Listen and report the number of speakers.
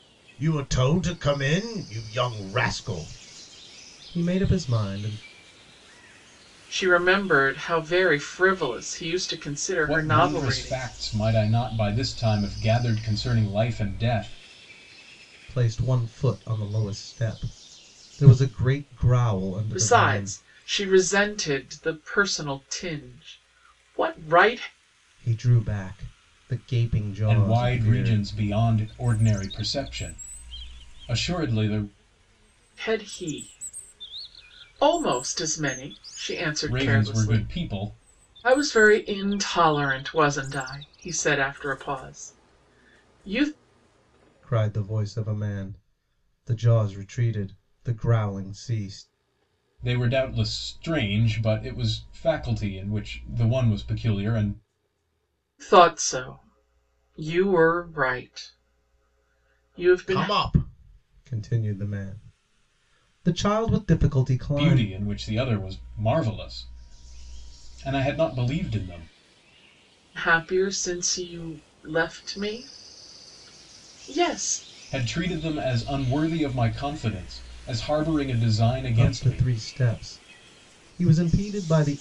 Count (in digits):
3